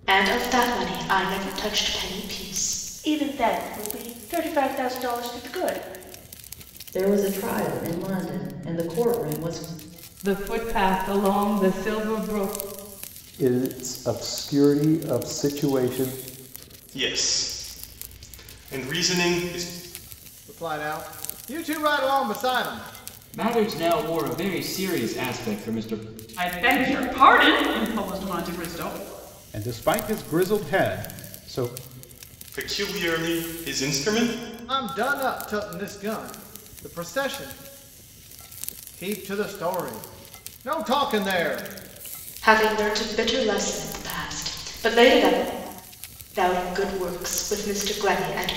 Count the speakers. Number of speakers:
10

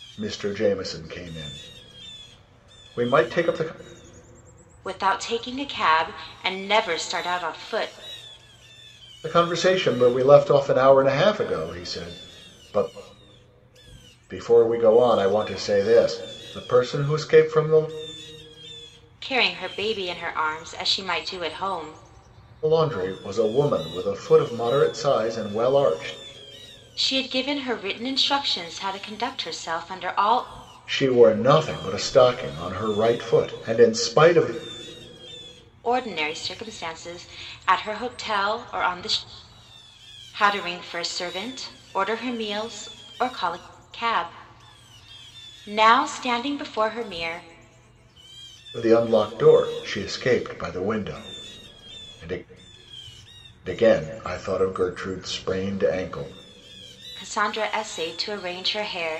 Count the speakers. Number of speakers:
2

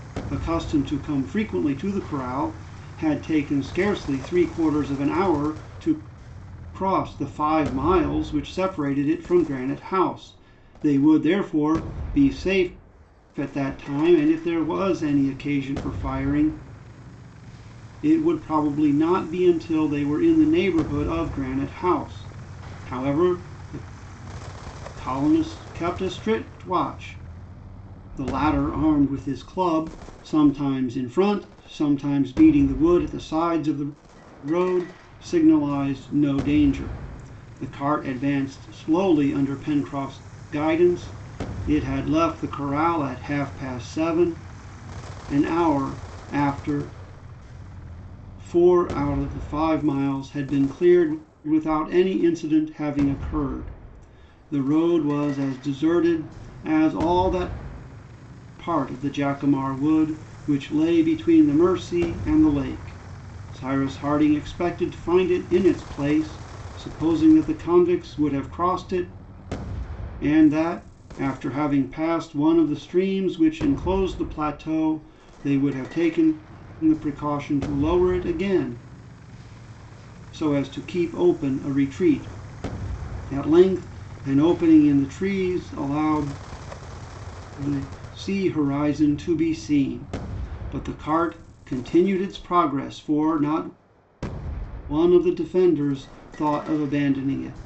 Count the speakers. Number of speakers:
1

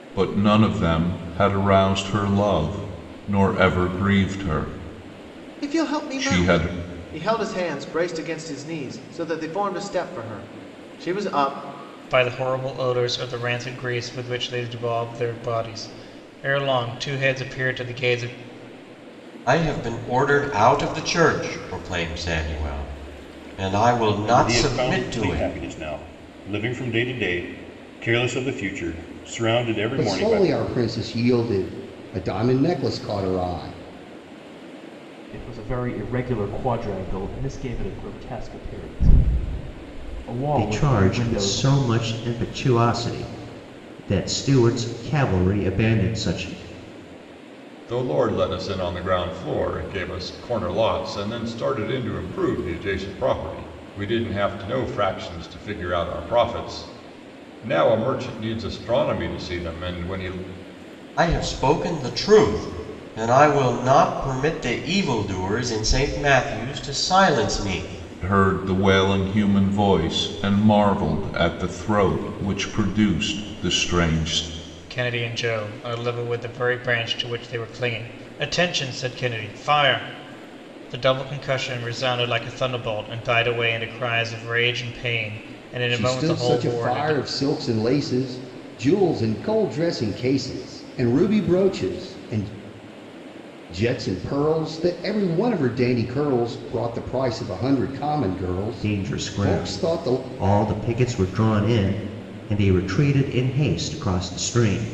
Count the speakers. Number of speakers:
9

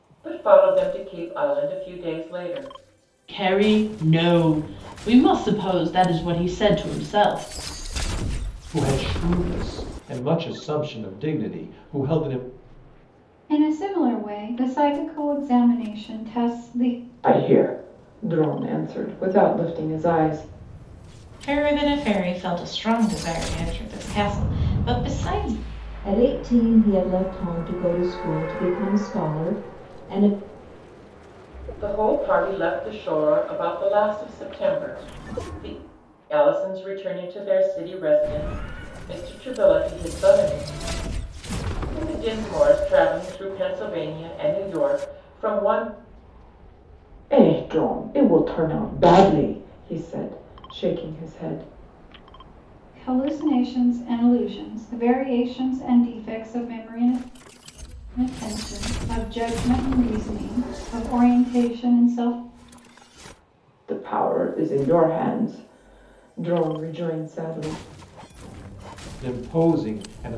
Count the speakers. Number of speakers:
7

